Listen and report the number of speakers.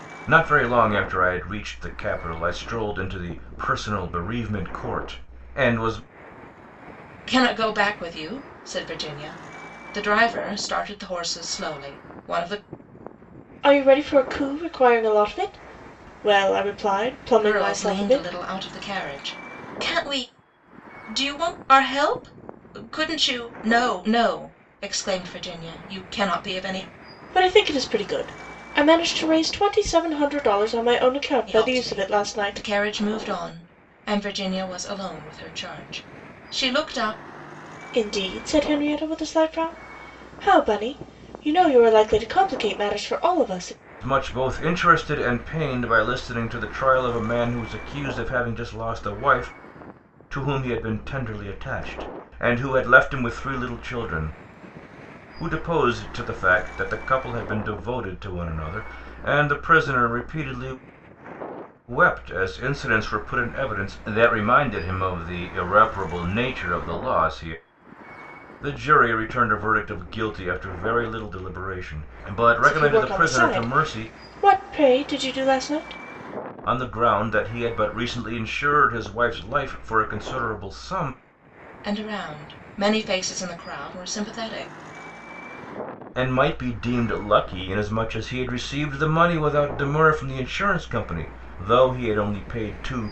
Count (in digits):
3